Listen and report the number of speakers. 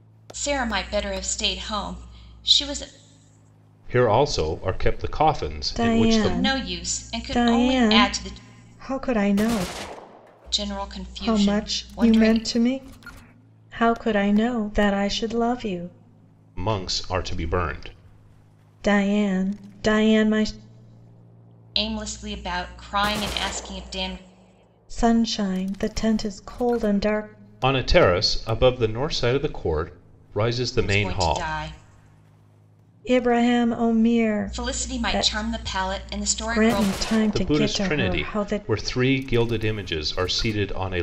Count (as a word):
three